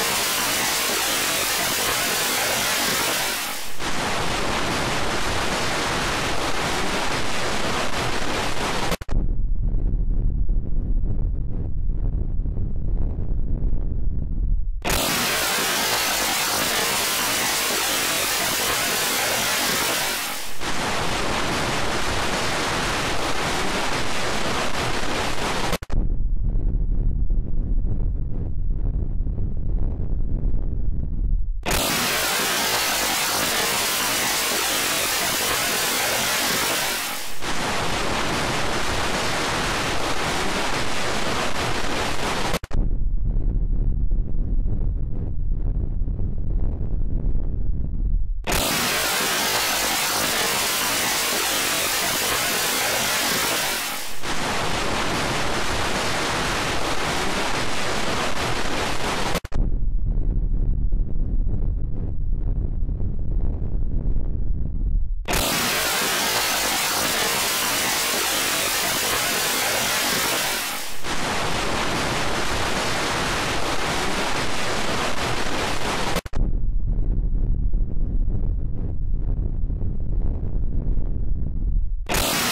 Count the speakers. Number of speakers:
zero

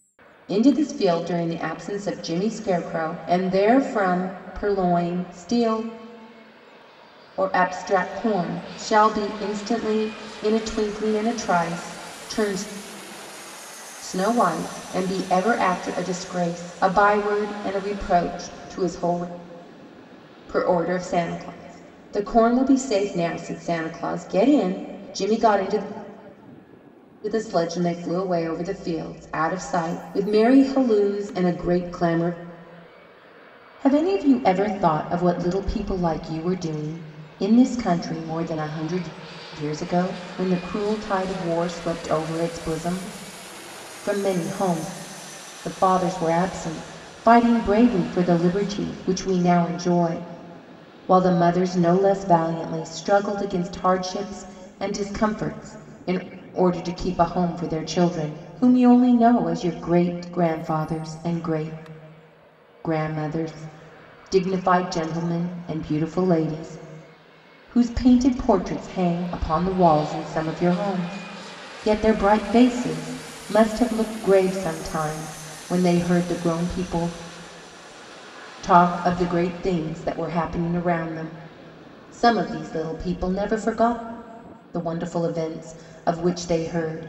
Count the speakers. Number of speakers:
one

